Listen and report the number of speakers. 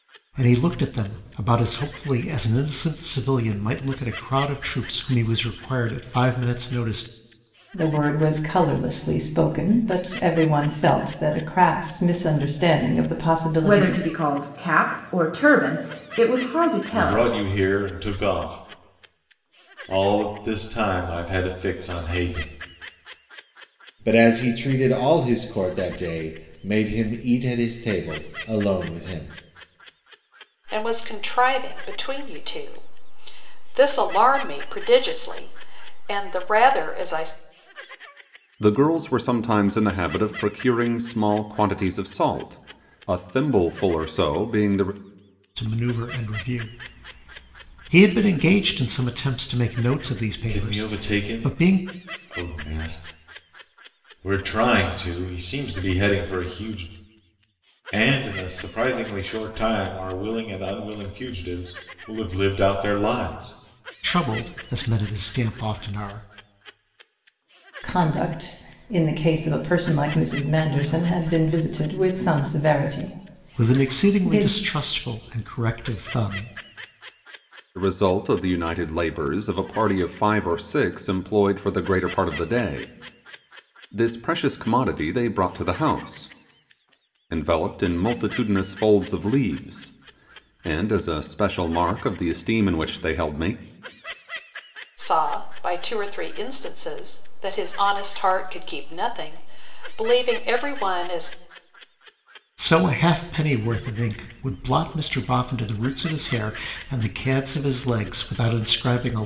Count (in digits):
7